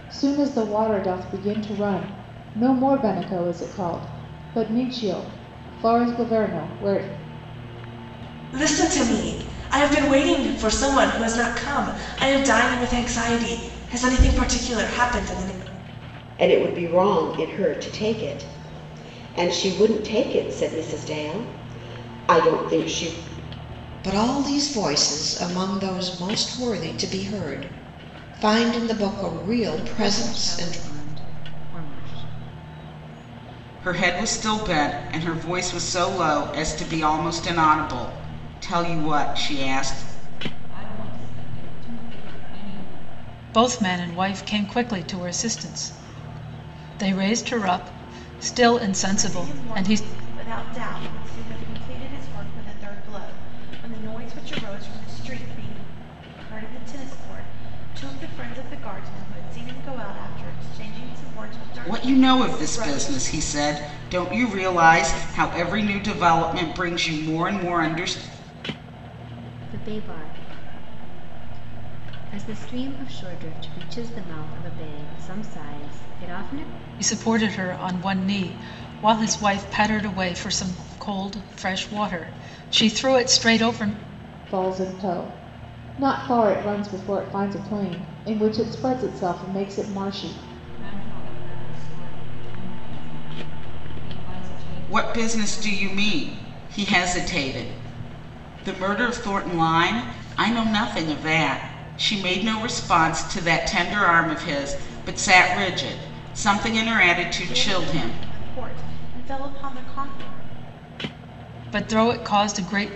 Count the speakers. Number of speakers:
nine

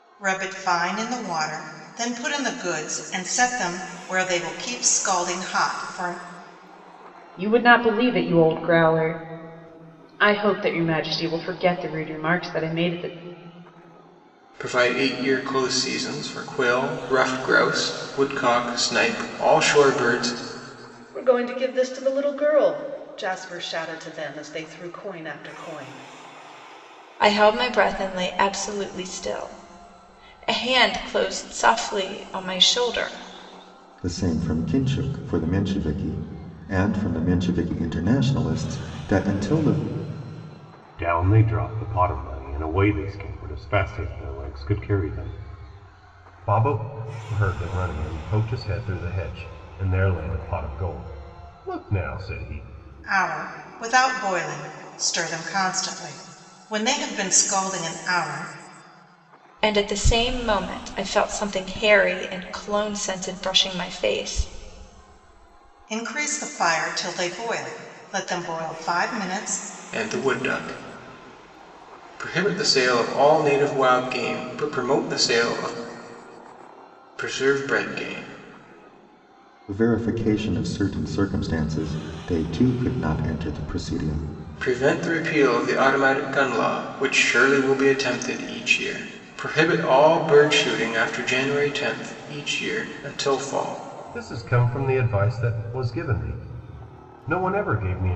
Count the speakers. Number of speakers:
seven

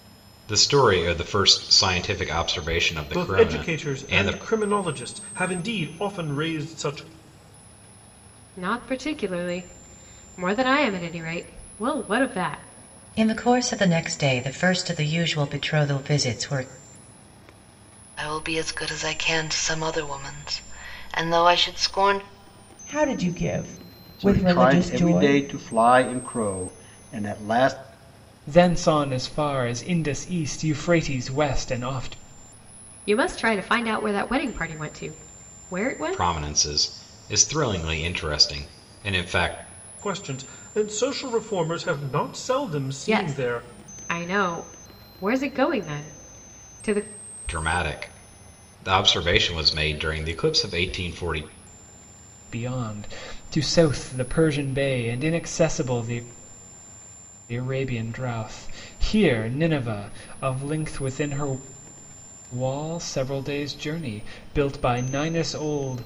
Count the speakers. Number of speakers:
eight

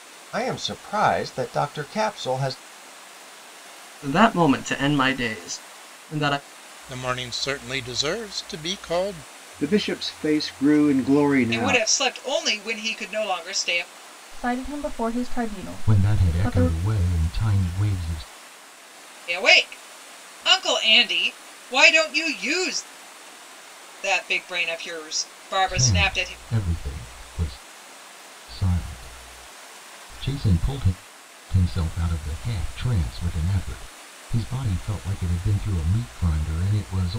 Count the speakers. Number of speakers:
seven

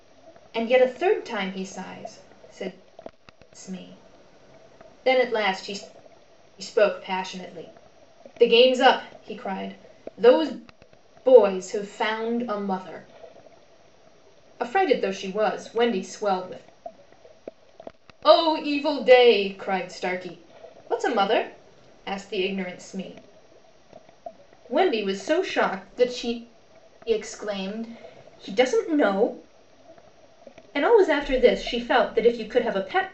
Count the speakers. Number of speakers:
one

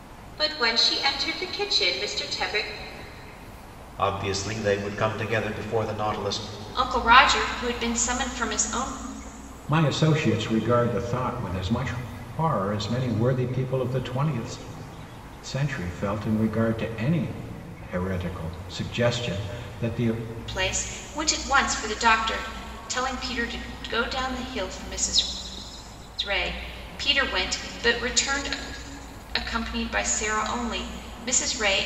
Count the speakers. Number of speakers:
four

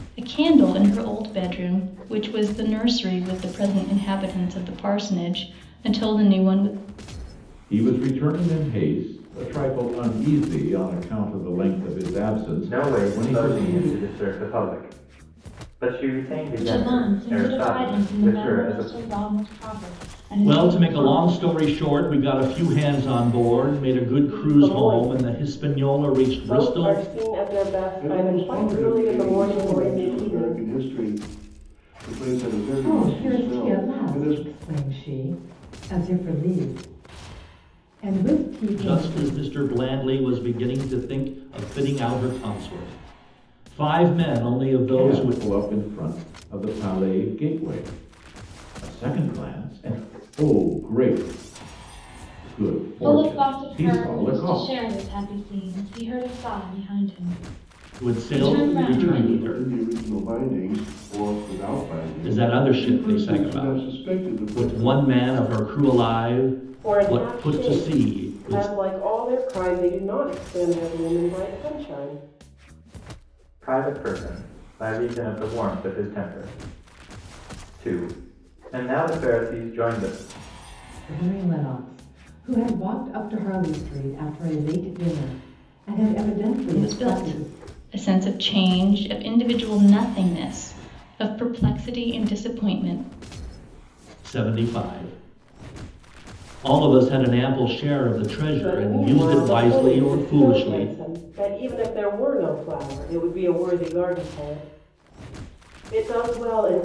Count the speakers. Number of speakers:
eight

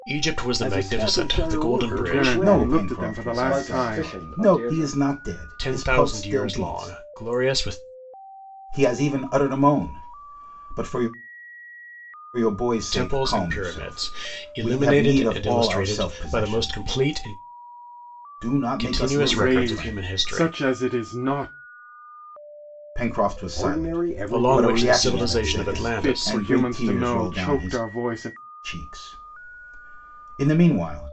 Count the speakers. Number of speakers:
five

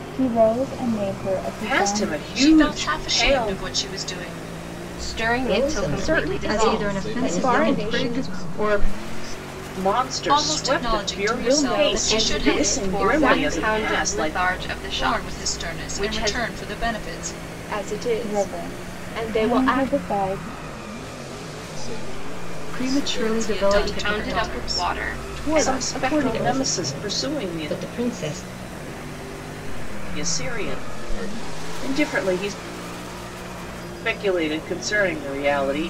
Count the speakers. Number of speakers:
eight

